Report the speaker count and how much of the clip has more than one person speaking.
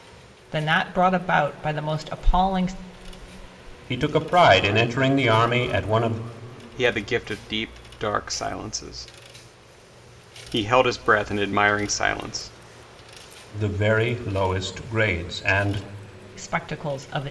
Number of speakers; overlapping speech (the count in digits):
3, no overlap